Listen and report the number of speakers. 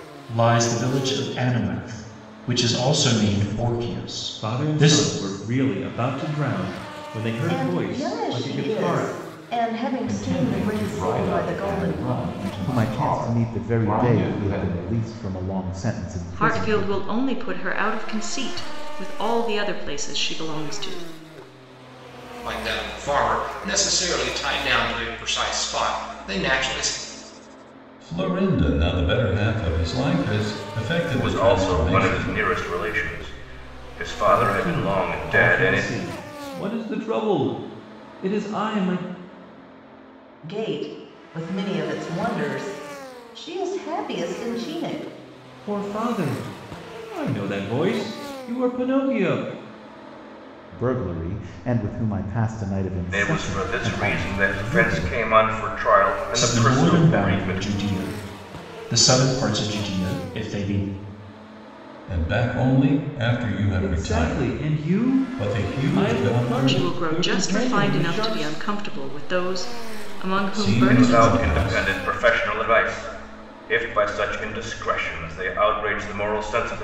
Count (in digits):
9